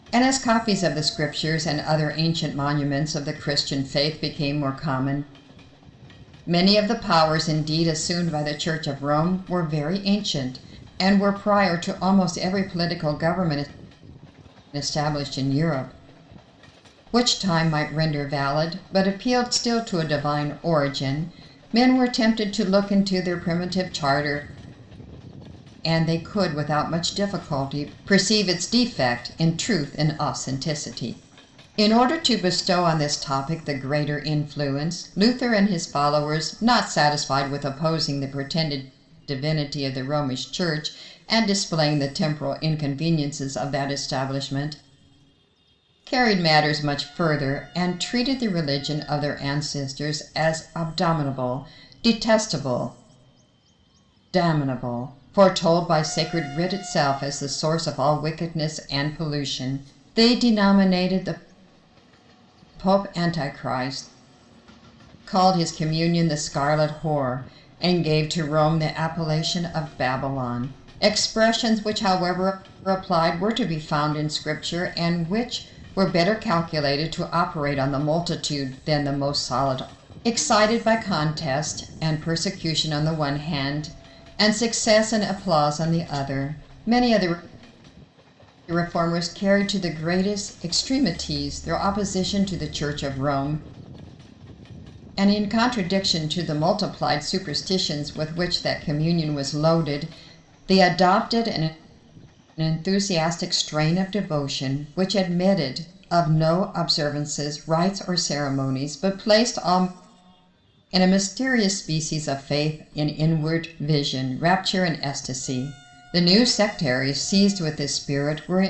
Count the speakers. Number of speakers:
one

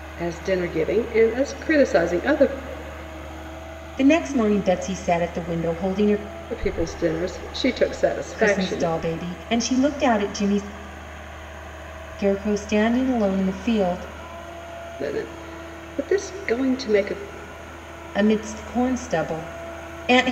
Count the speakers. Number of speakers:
two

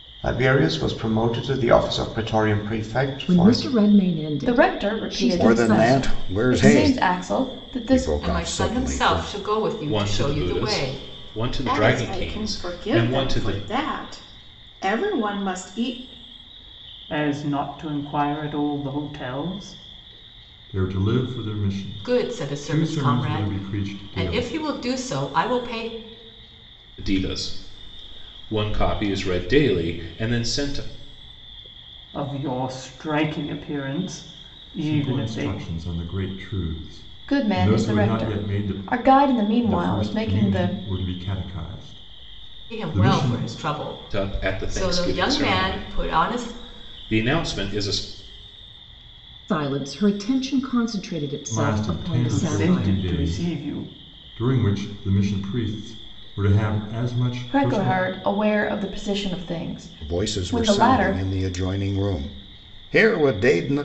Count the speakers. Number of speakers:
nine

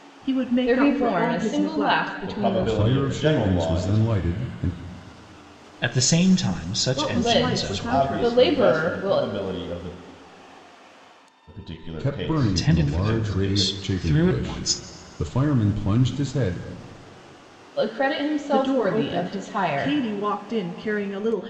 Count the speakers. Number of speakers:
five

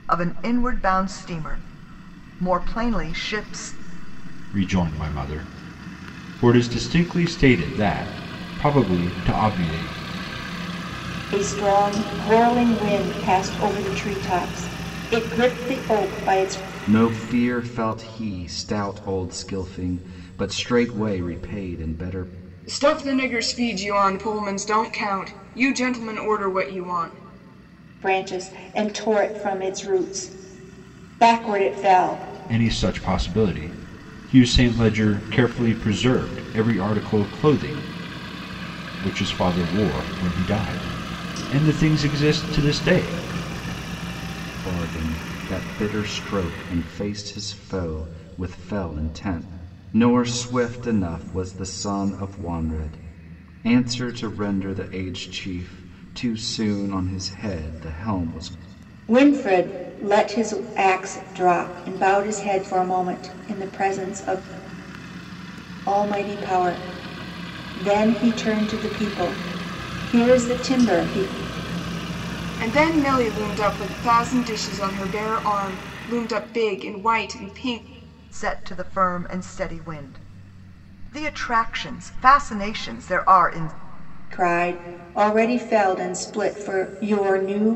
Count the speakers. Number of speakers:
five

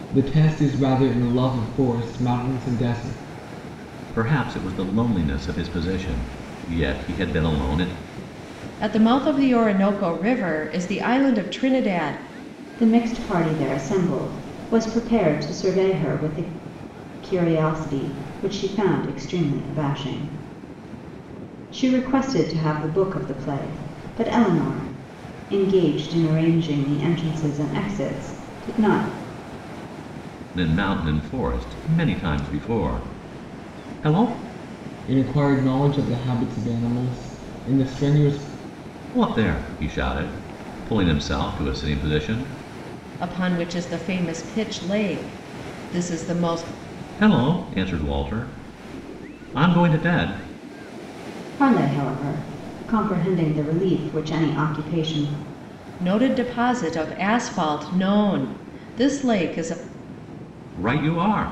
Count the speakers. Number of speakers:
four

